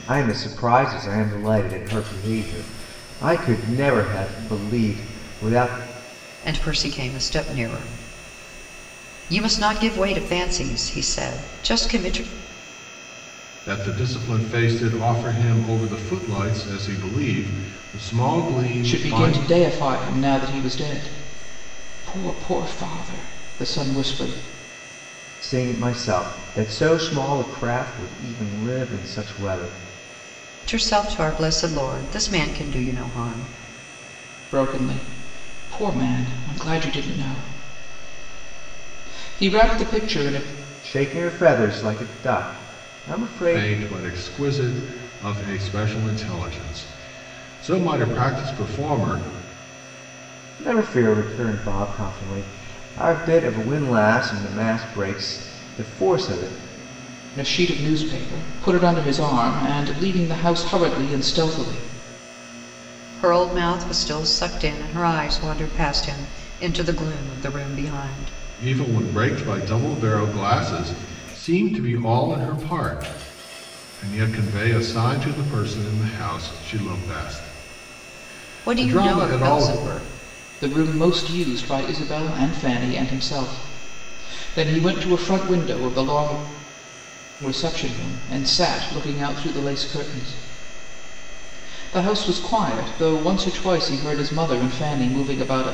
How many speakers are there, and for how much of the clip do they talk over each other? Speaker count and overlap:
four, about 2%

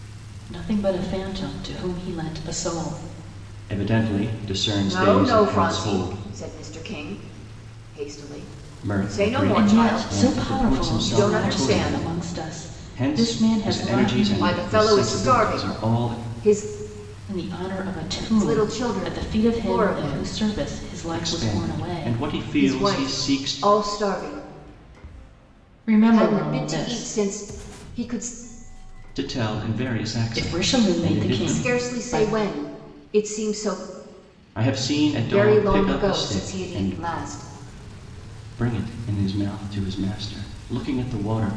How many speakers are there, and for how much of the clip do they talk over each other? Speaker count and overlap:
three, about 42%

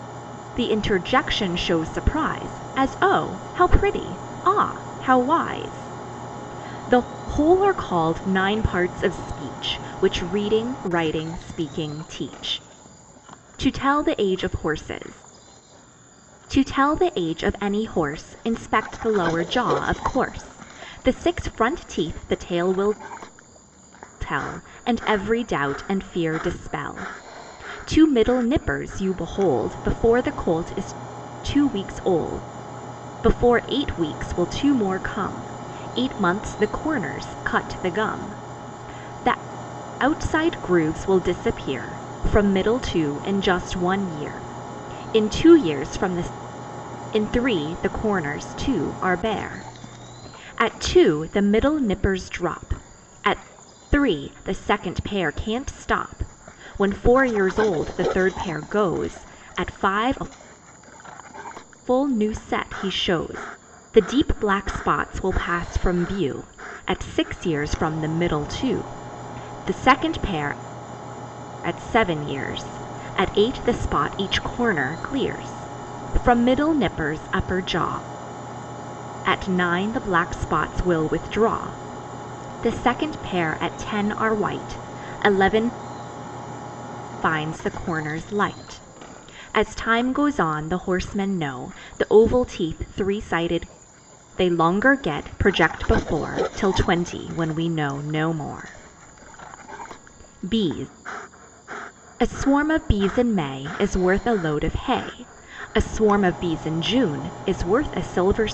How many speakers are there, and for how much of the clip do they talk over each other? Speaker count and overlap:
one, no overlap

